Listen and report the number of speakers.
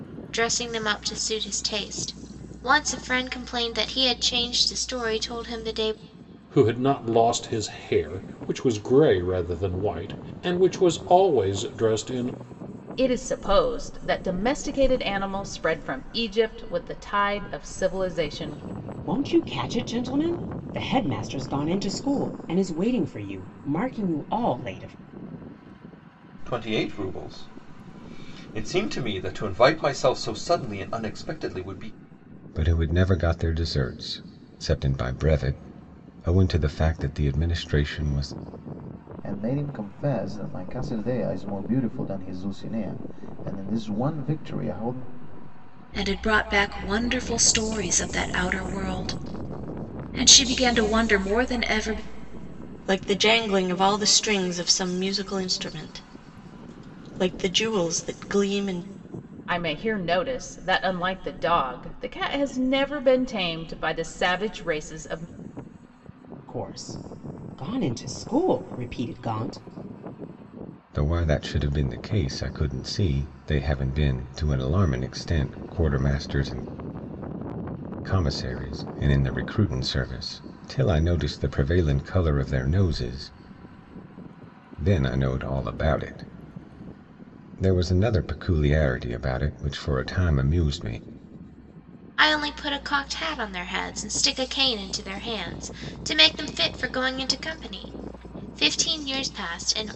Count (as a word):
nine